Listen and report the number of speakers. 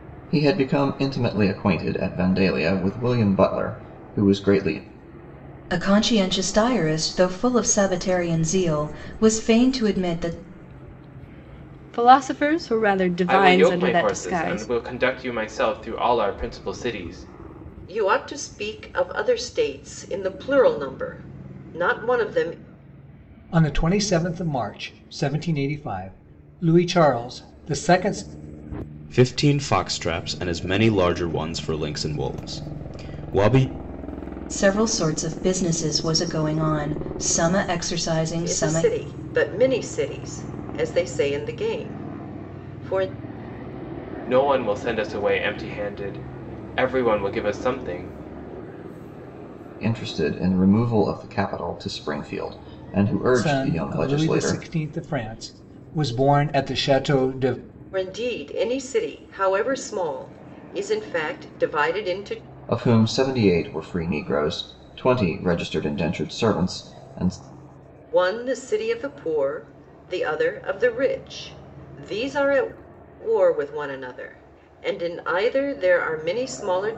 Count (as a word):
seven